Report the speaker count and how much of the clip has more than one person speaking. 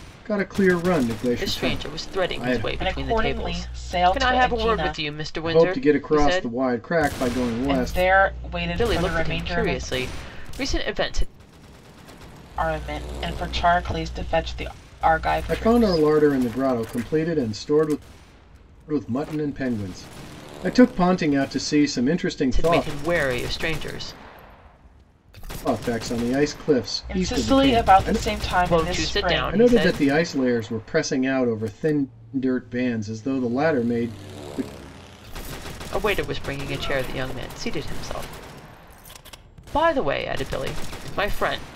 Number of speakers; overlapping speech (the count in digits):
3, about 22%